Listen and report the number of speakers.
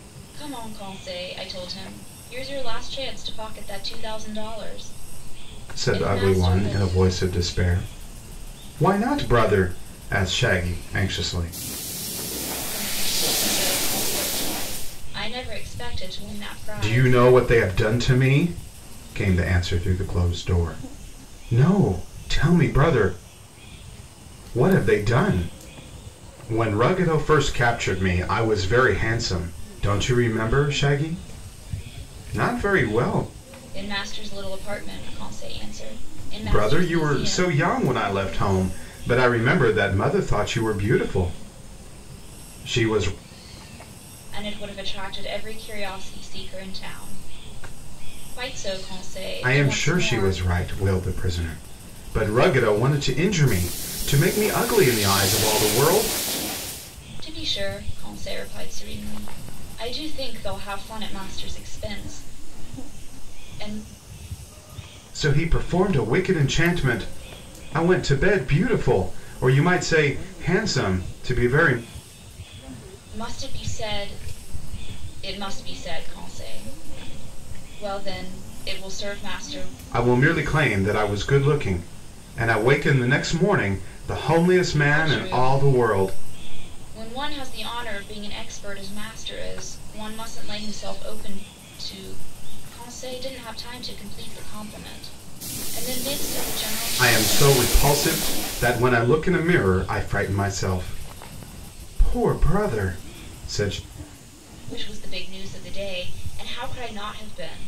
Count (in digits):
2